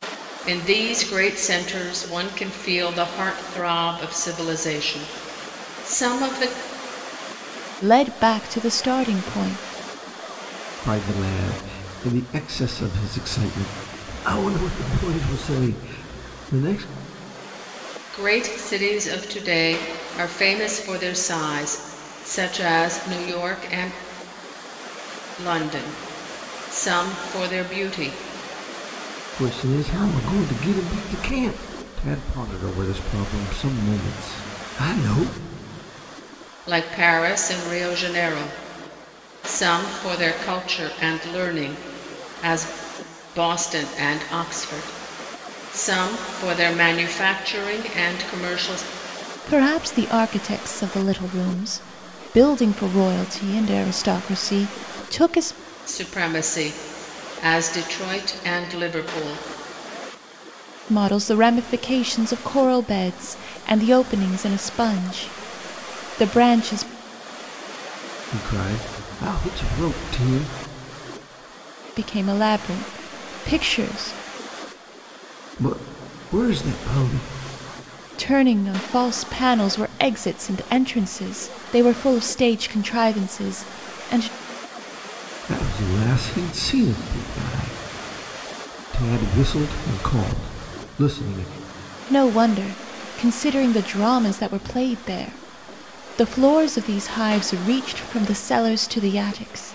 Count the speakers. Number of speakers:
three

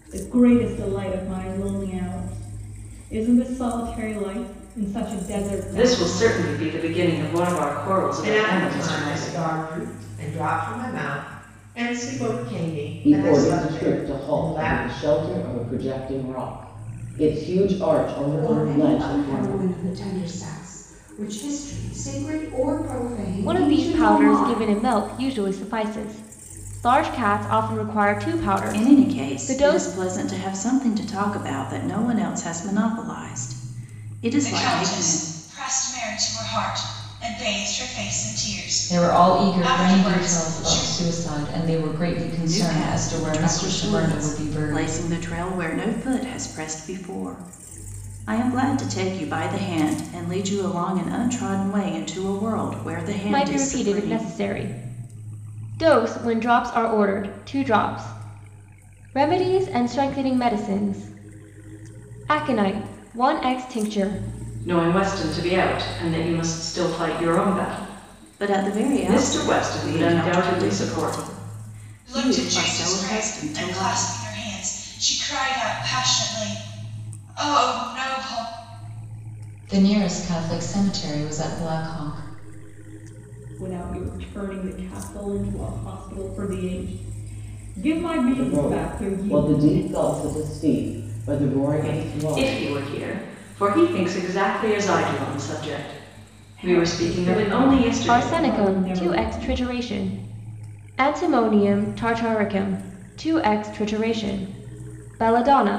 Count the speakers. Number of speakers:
nine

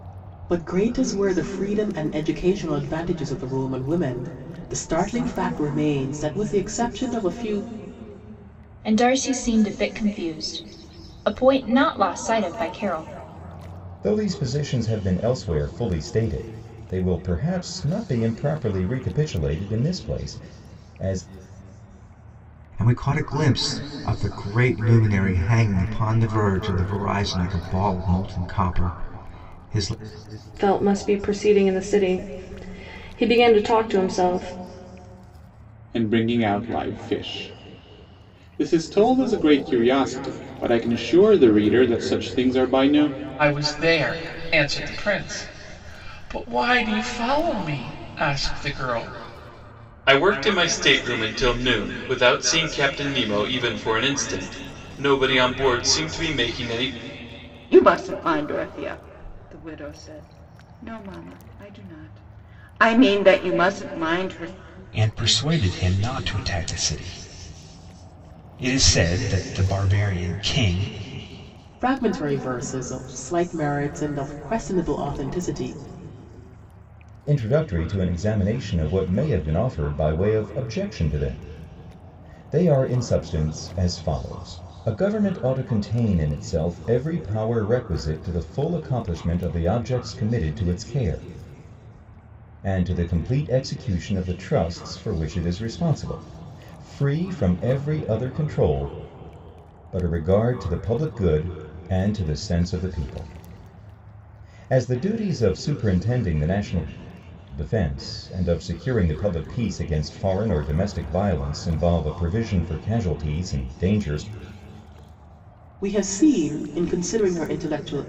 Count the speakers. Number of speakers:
ten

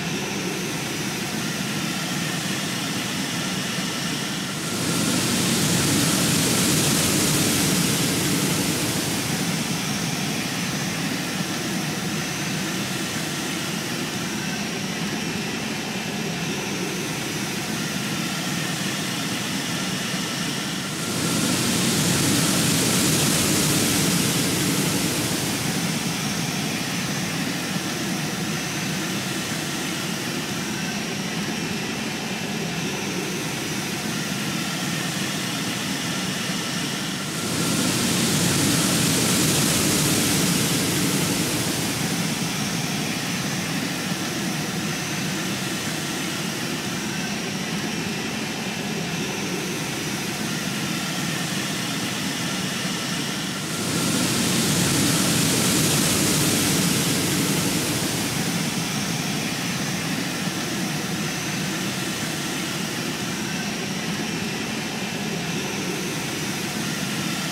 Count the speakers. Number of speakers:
zero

